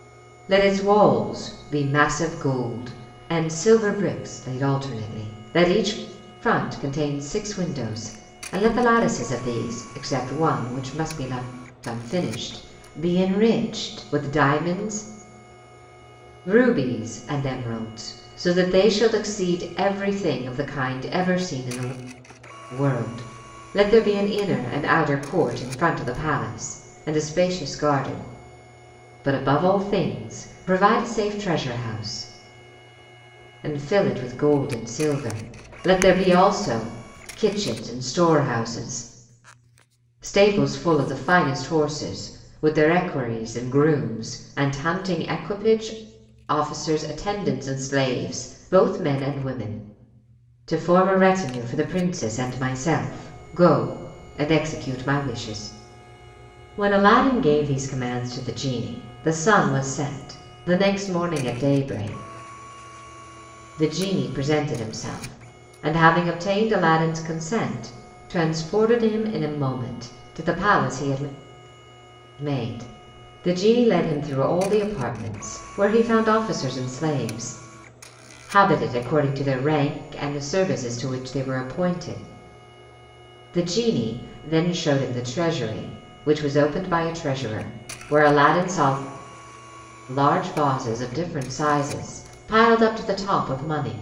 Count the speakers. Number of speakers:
1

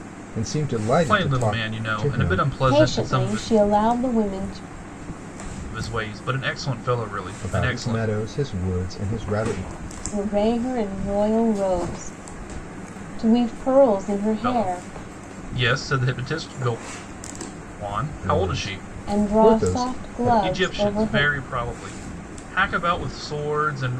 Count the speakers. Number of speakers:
3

